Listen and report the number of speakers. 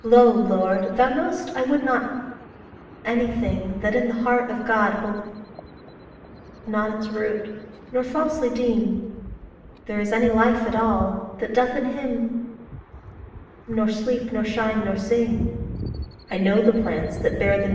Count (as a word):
one